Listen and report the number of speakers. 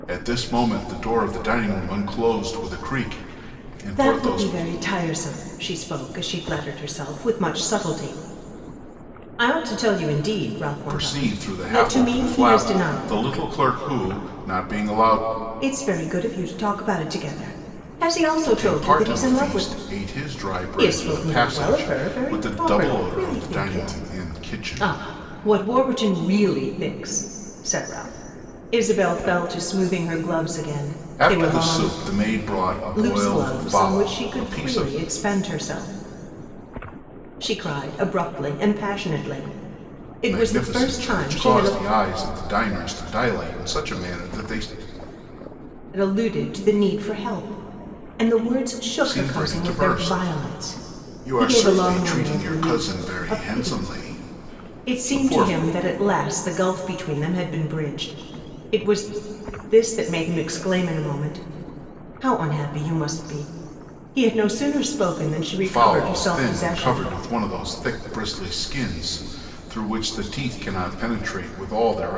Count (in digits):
2